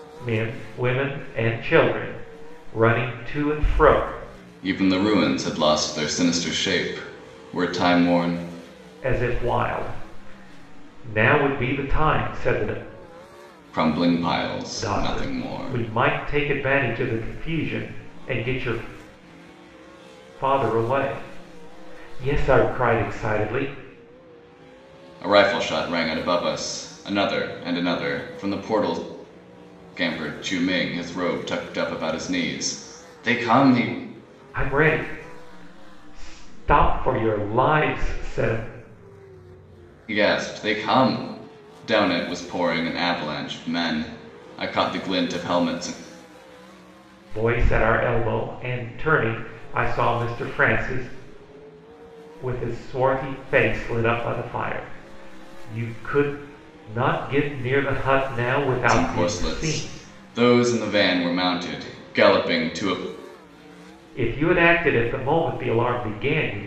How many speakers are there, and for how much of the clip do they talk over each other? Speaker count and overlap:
two, about 3%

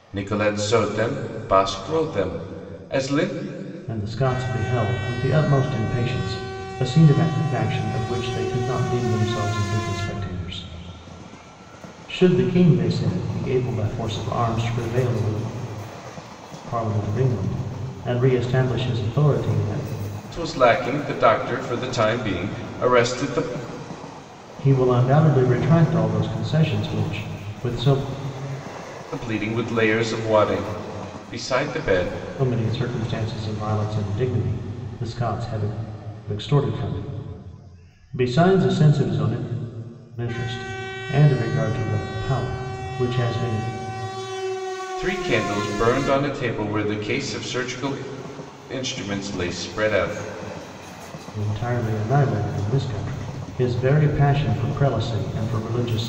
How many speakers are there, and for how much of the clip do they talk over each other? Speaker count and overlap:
two, no overlap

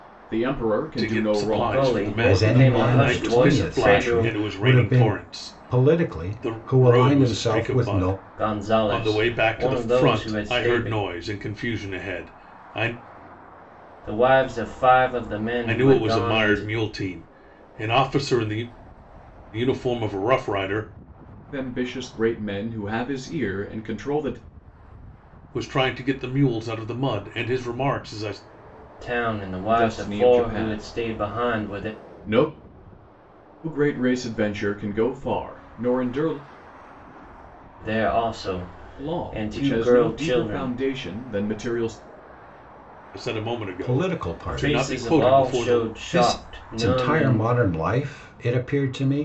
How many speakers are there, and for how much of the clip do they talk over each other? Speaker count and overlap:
four, about 36%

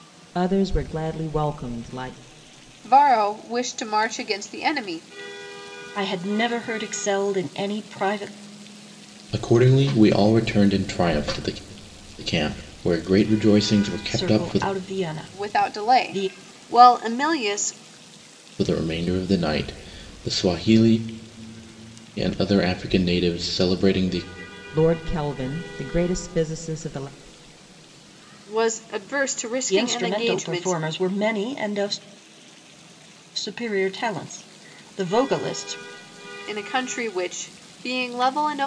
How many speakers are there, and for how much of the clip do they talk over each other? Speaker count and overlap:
four, about 7%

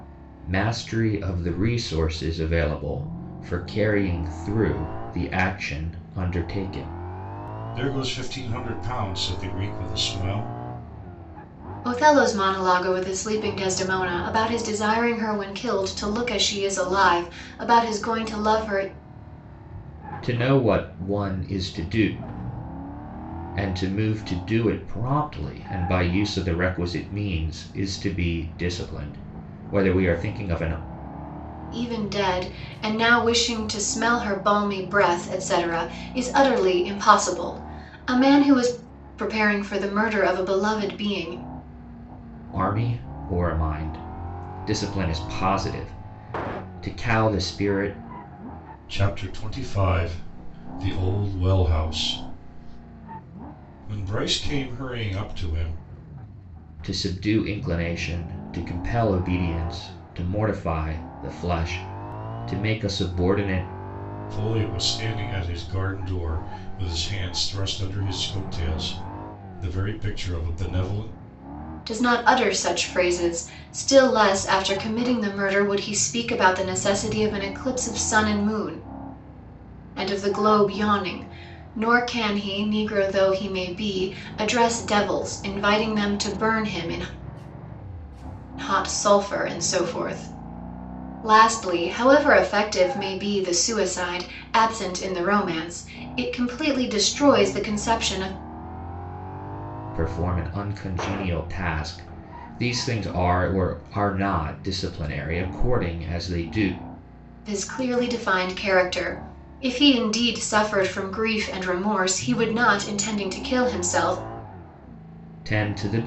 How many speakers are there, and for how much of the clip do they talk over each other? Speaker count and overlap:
three, no overlap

